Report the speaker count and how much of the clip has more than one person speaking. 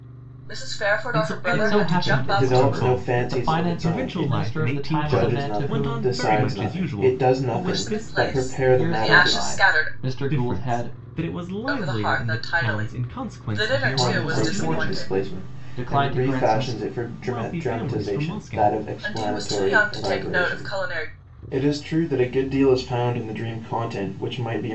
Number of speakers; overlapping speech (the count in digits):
4, about 71%